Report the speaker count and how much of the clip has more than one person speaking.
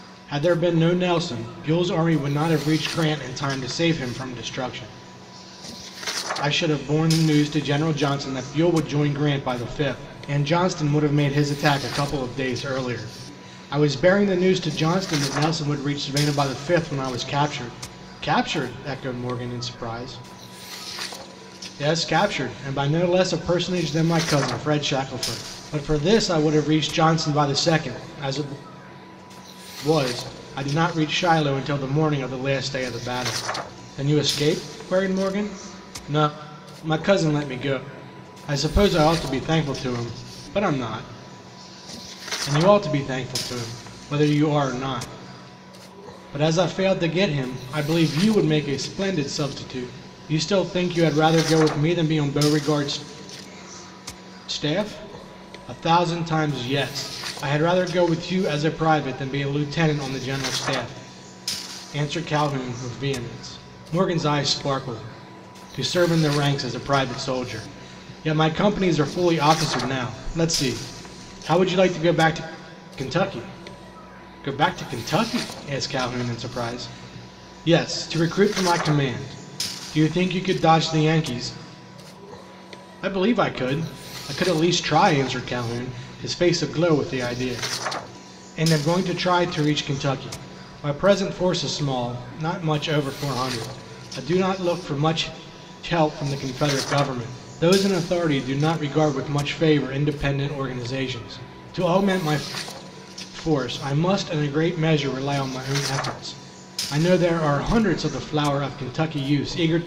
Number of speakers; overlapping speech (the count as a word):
one, no overlap